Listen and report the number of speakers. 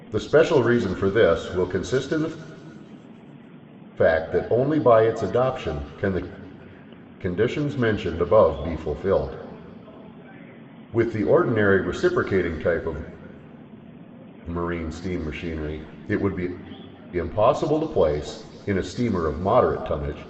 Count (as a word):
one